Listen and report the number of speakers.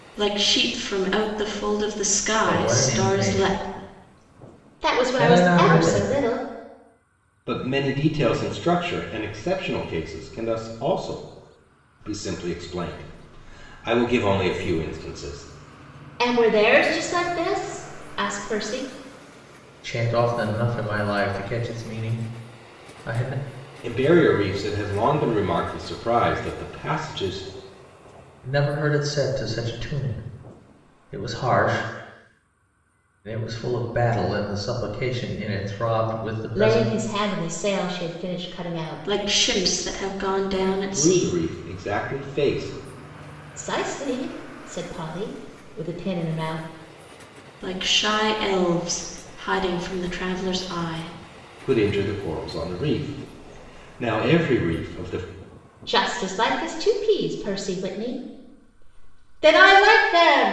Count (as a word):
four